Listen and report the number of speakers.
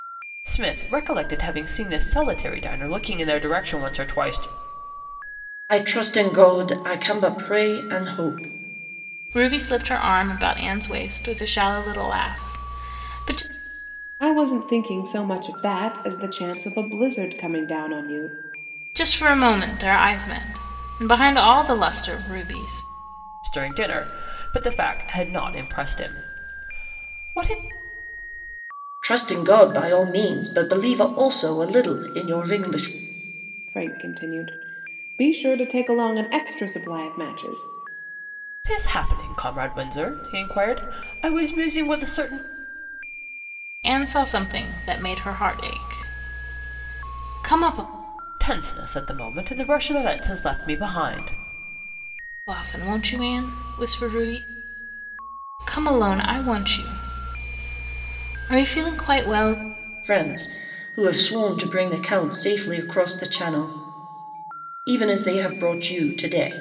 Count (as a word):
four